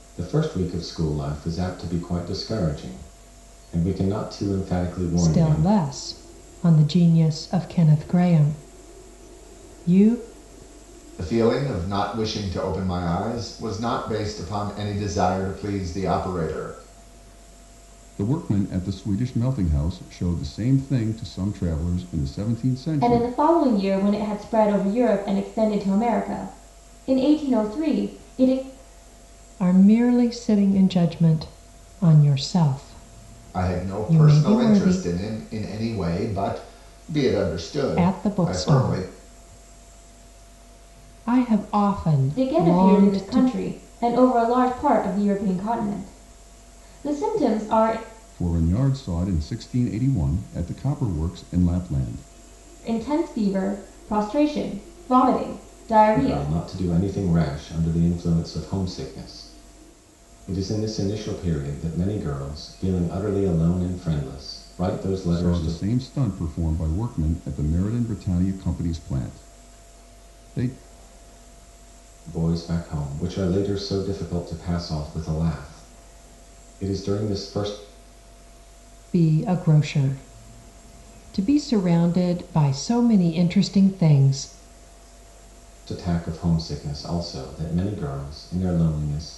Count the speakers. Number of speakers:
5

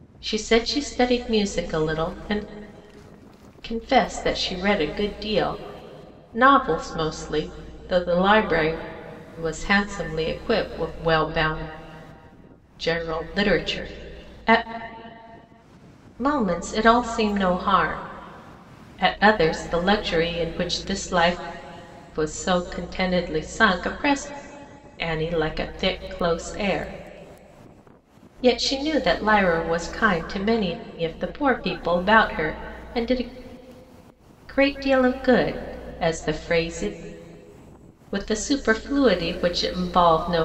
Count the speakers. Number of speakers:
1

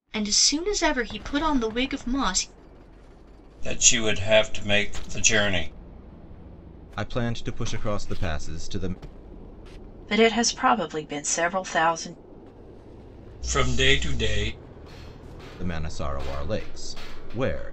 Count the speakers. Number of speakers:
4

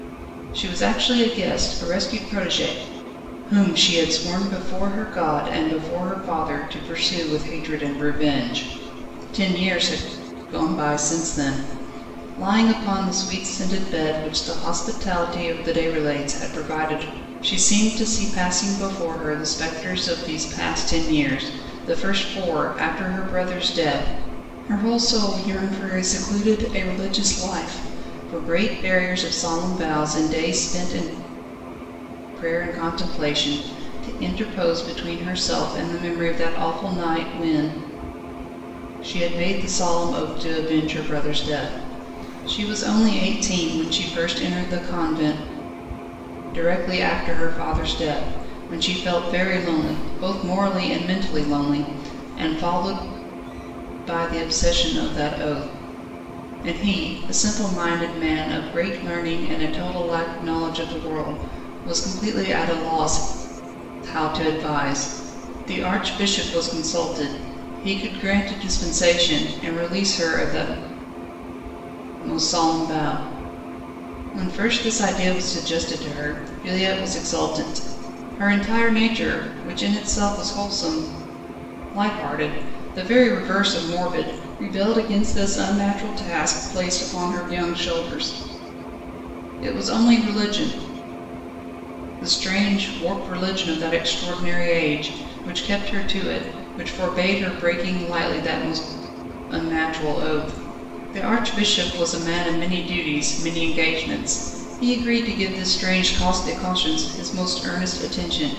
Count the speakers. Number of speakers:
1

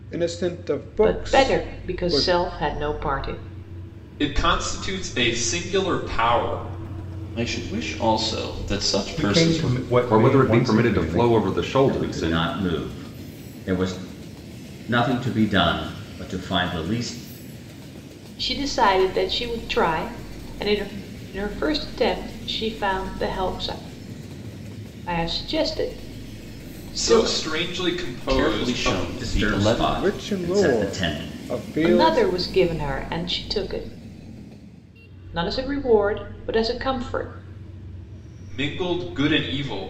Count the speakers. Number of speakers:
7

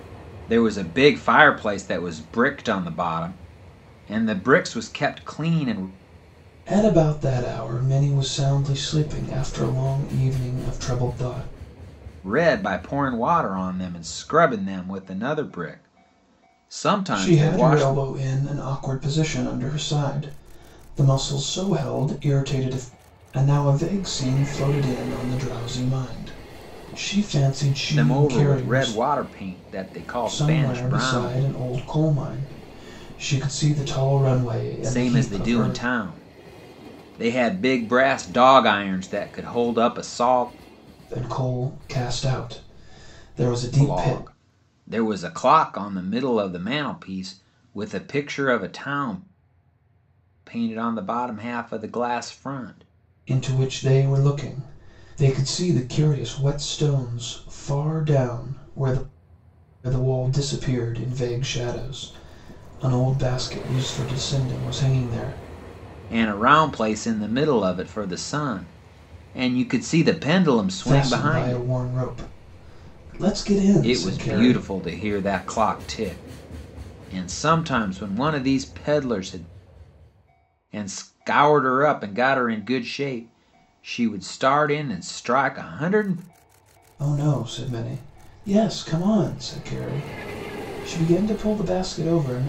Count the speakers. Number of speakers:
2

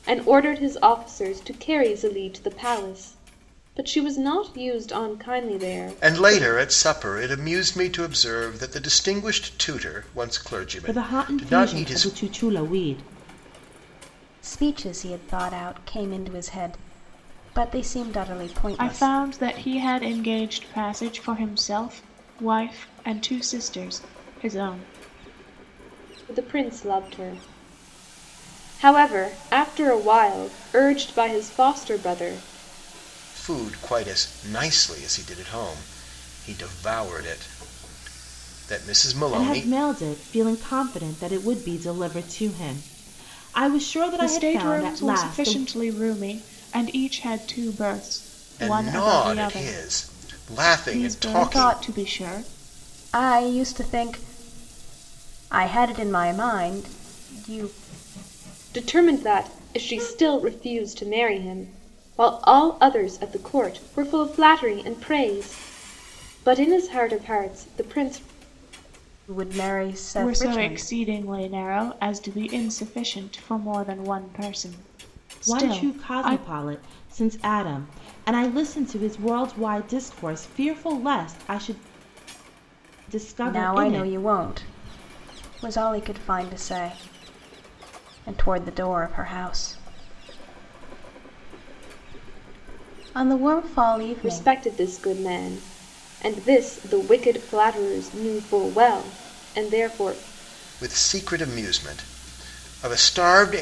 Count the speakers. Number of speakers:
5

